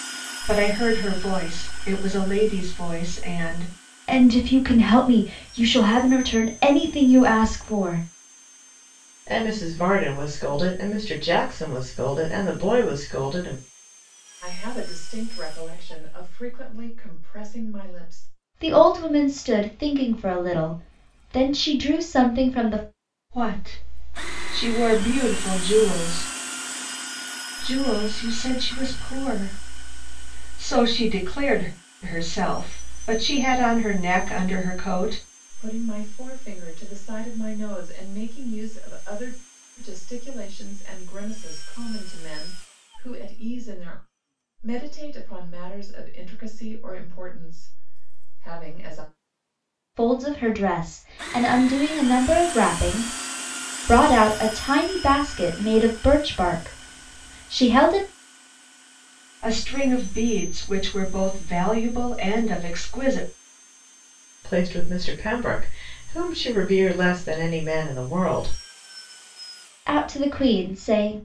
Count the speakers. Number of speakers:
4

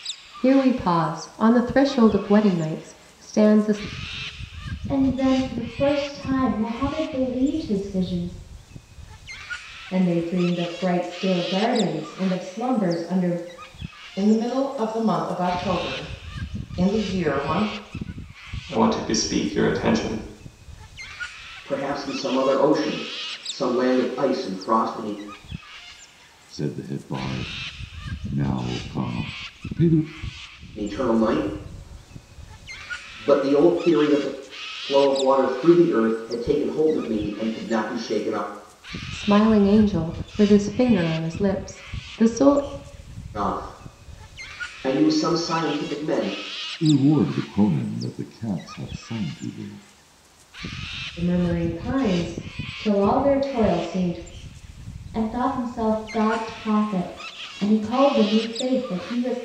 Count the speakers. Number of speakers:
7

